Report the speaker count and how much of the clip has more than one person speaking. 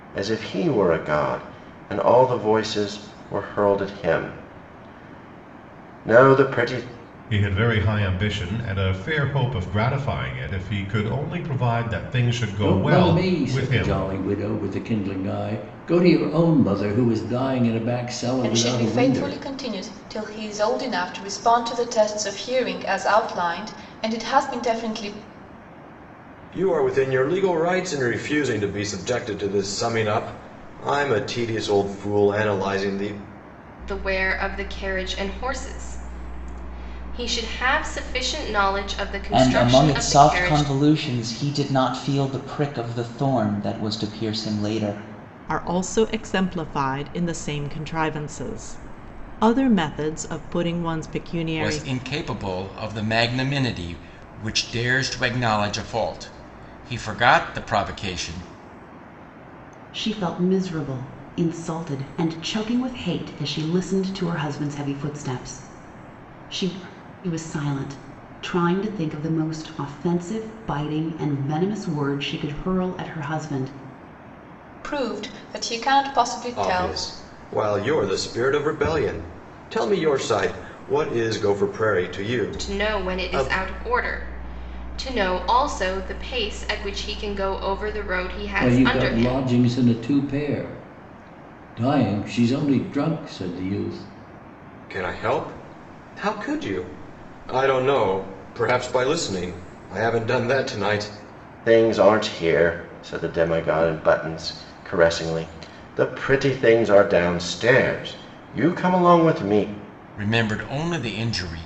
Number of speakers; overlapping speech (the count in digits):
10, about 6%